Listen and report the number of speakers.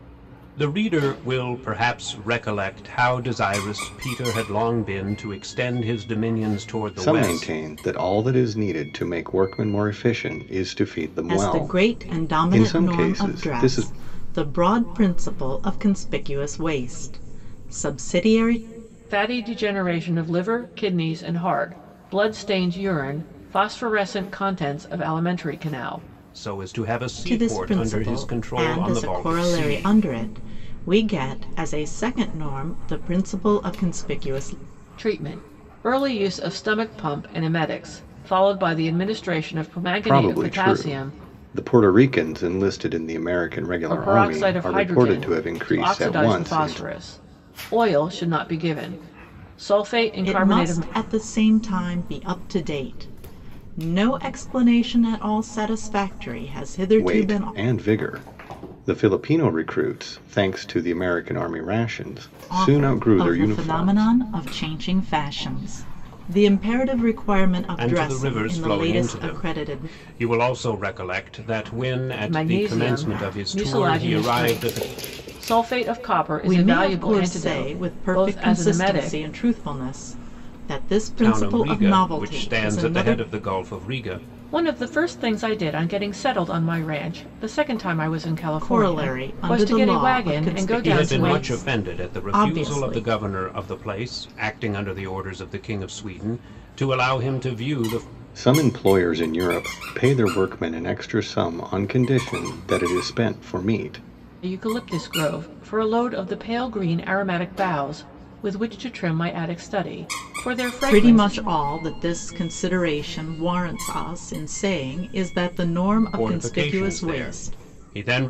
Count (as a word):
four